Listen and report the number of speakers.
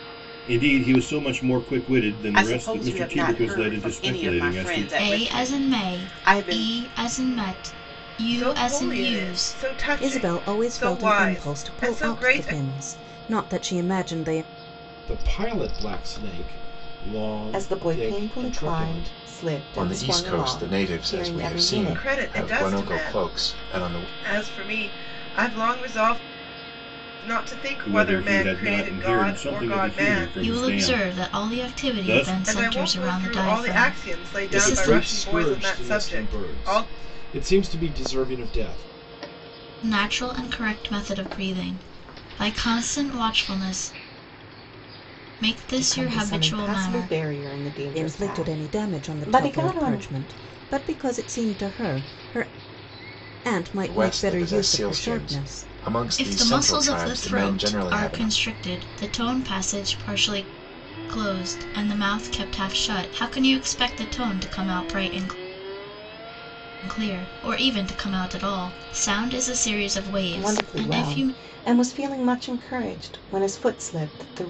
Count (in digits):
8